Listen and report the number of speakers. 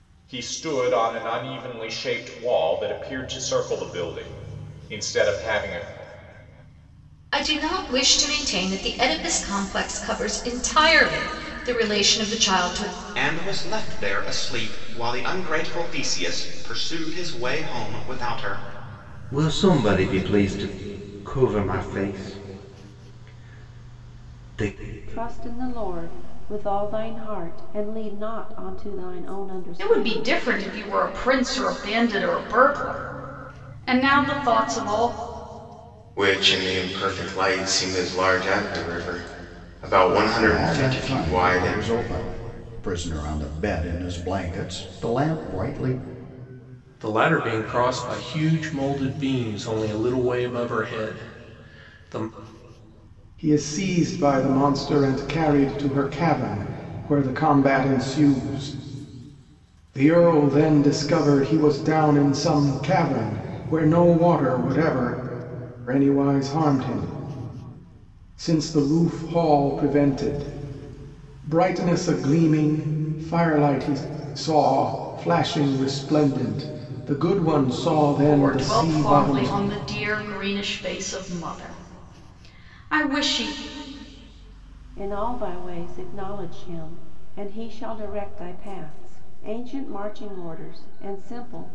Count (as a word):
ten